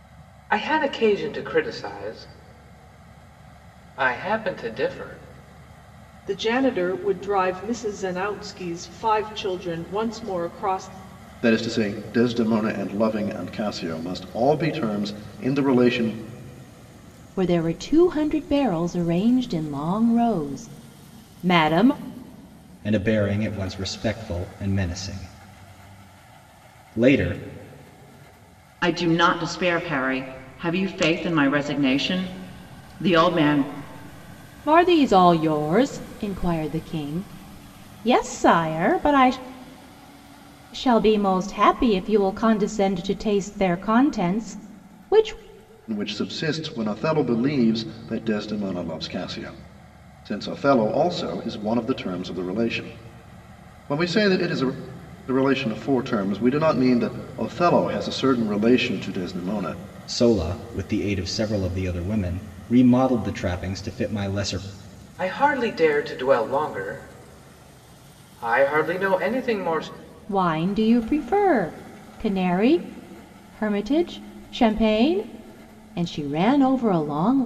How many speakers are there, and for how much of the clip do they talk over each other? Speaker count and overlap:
six, no overlap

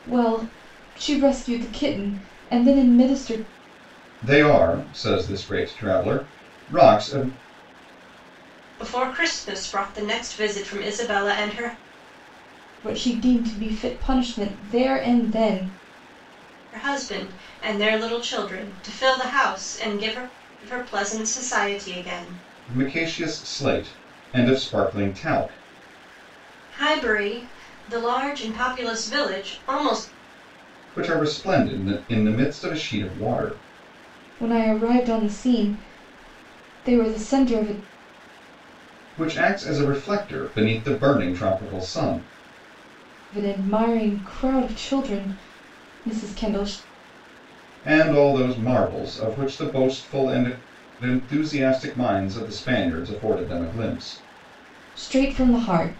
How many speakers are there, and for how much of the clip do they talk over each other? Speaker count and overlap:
three, no overlap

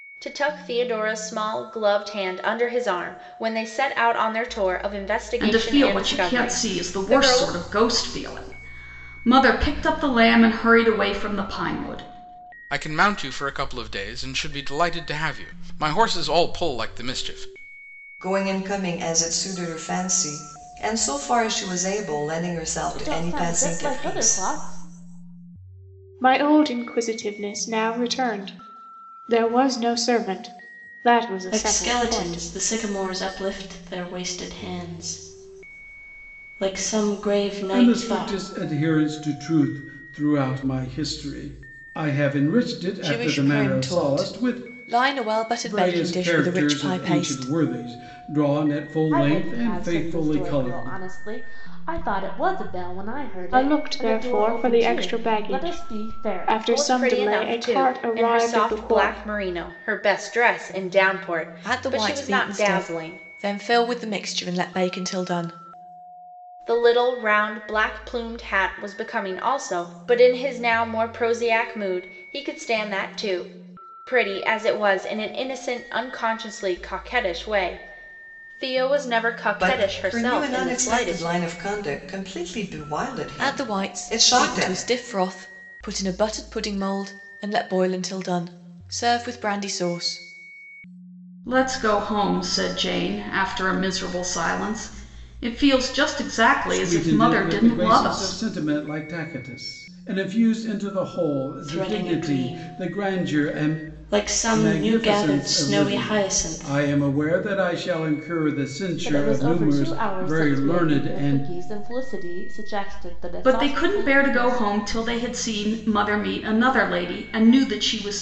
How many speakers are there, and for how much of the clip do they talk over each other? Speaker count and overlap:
nine, about 27%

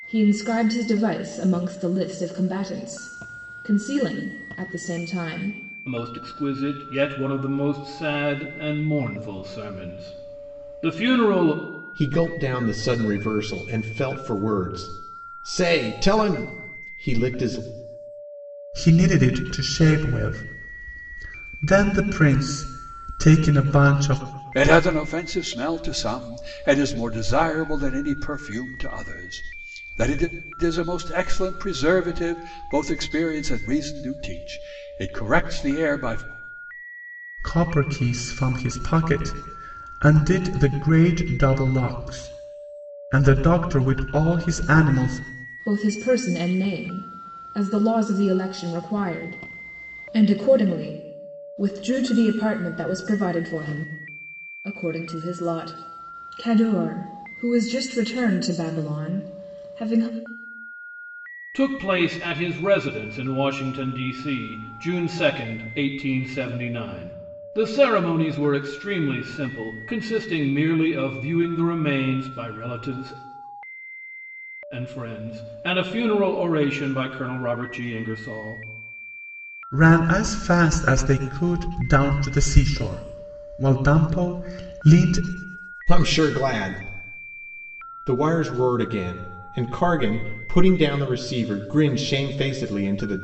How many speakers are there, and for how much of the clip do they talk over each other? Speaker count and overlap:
five, no overlap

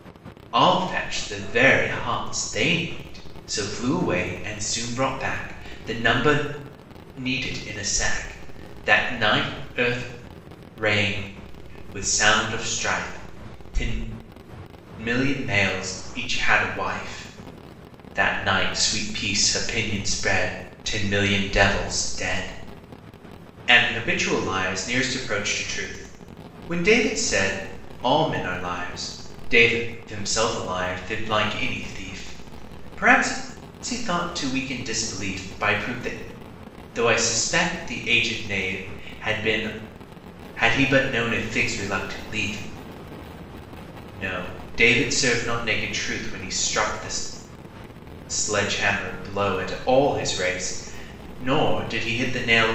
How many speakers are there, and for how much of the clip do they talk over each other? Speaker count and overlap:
one, no overlap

